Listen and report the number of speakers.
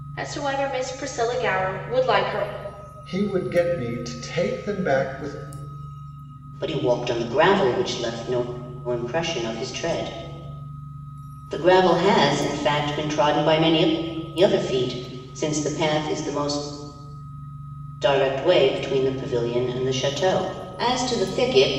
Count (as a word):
three